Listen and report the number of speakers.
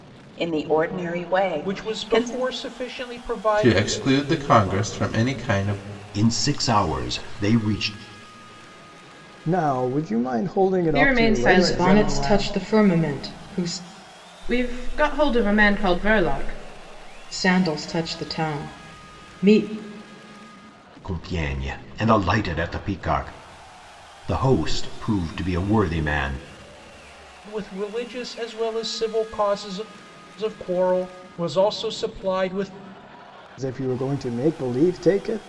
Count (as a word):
seven